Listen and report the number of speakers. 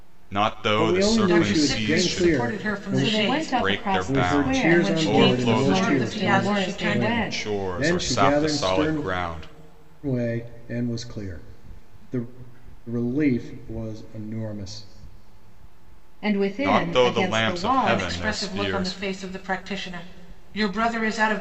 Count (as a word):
four